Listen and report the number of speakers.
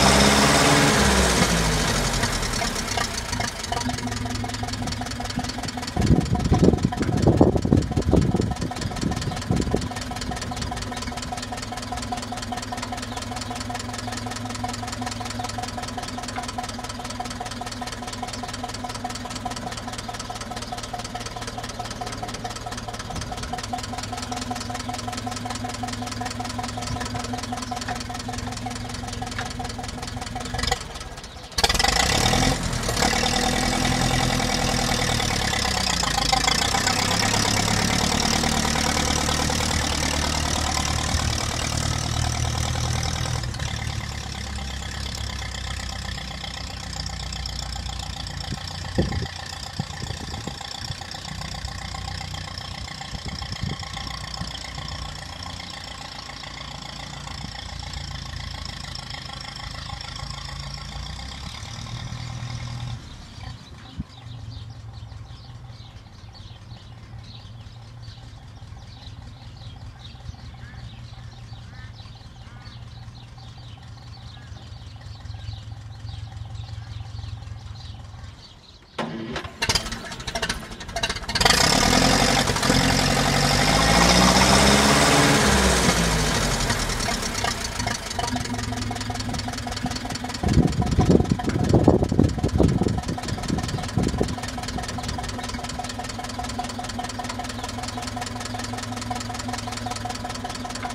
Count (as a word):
zero